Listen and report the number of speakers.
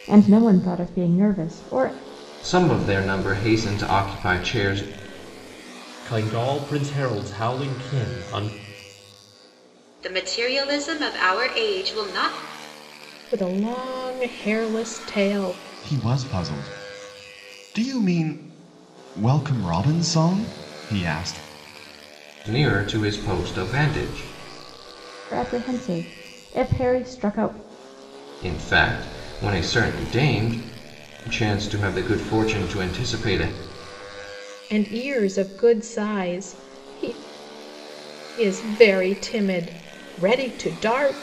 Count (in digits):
6